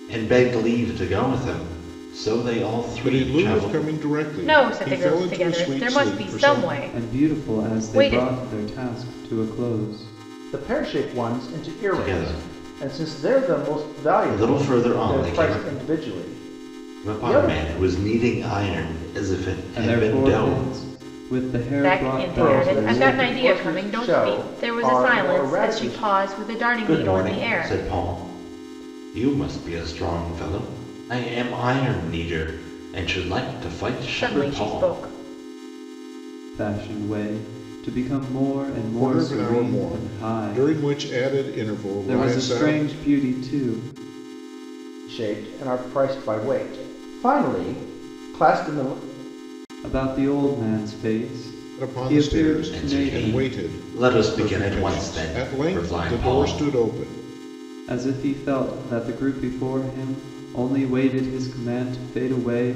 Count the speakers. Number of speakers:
5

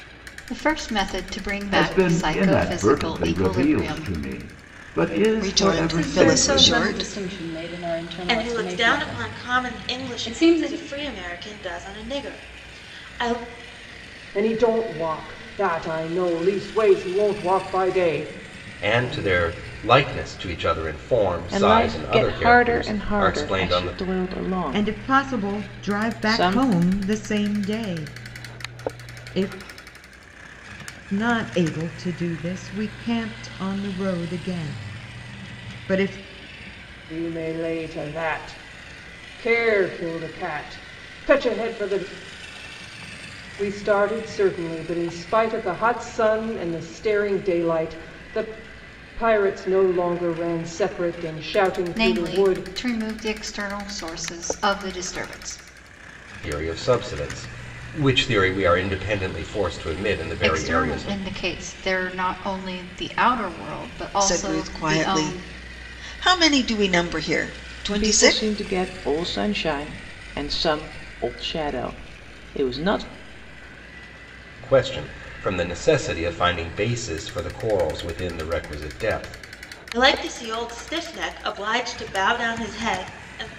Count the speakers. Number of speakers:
9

